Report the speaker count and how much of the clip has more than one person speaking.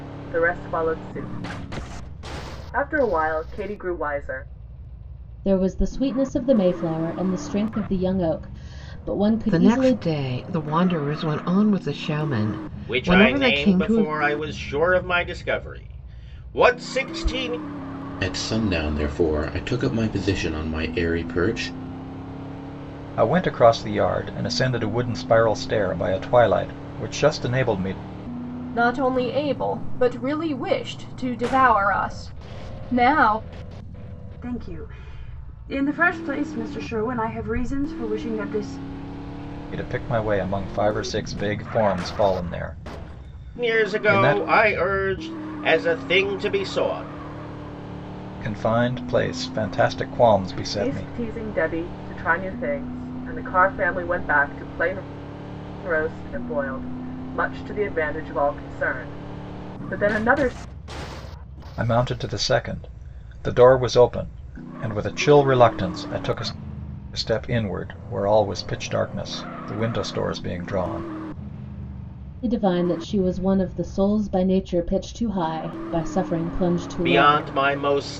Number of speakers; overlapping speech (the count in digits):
8, about 5%